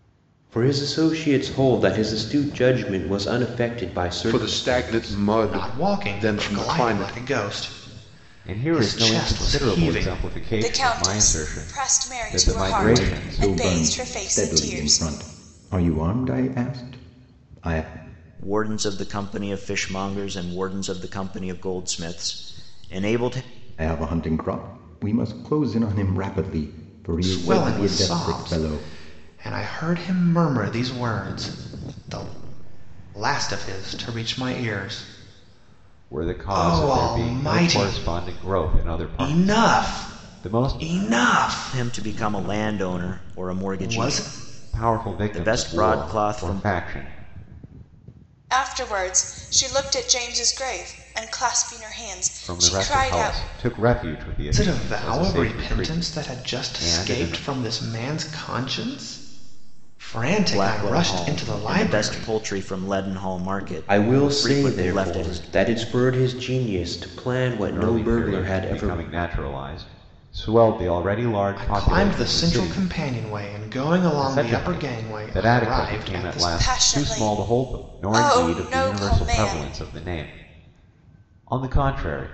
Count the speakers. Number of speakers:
7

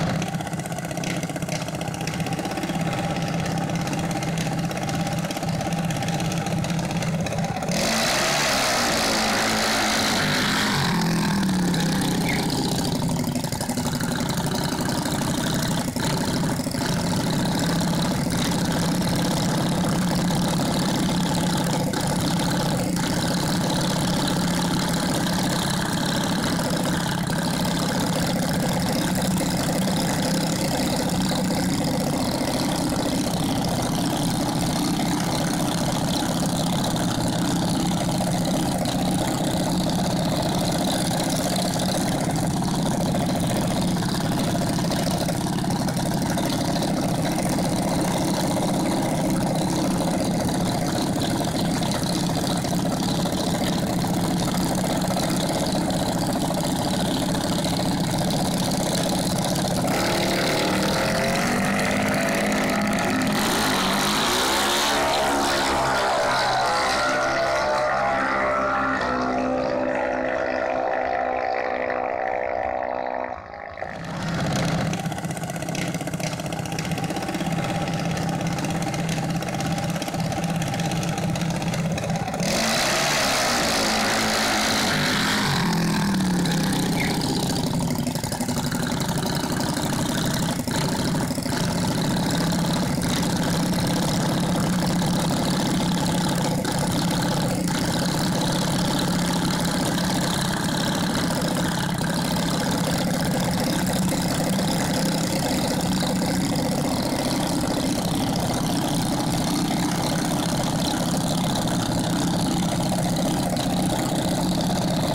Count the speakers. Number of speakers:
0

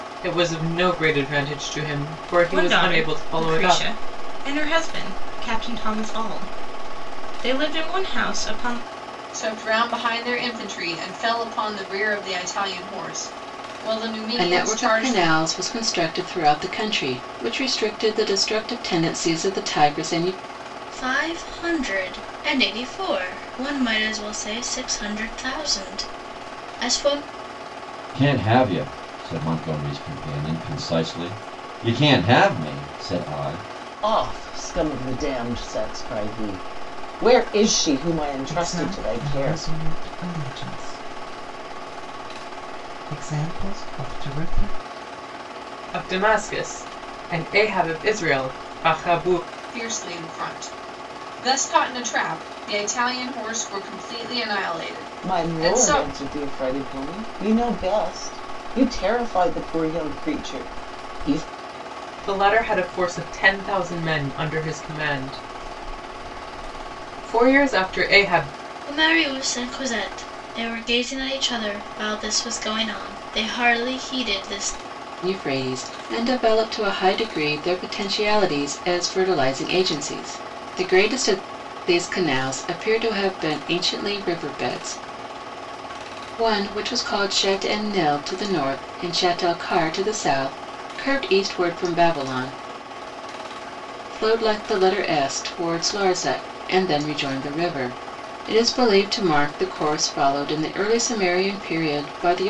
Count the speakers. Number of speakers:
8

